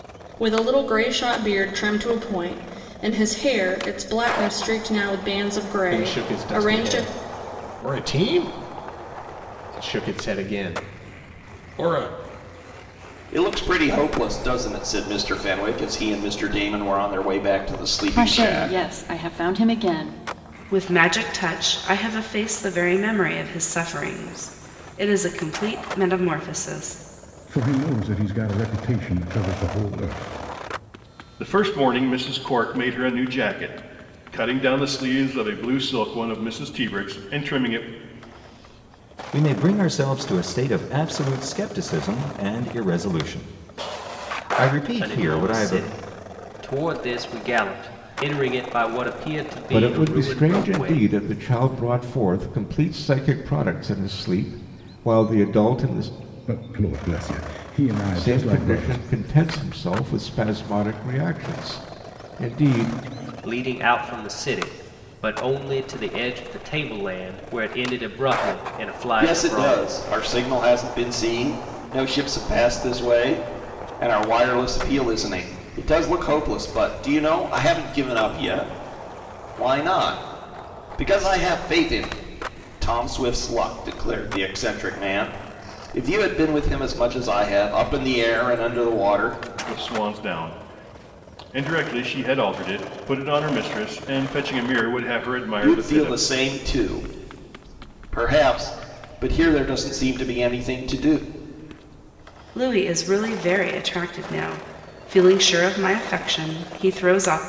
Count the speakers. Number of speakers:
ten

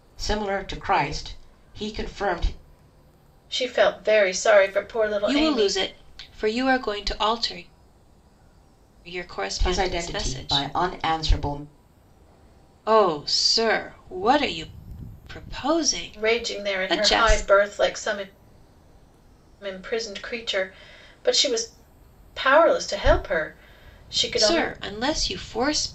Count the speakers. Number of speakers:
three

